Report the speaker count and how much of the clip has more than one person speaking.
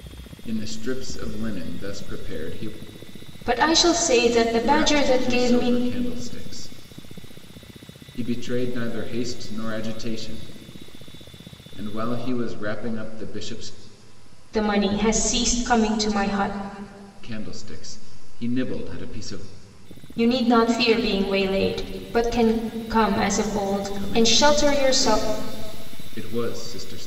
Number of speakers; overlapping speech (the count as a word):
two, about 9%